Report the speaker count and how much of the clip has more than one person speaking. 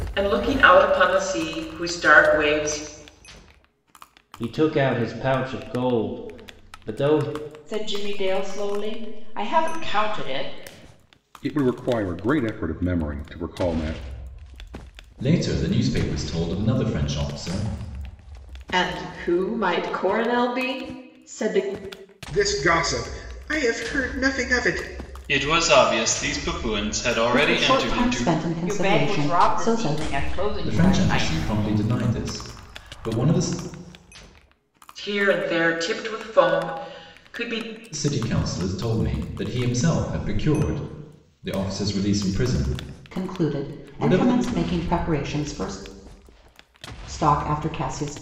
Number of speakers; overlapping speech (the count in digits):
9, about 9%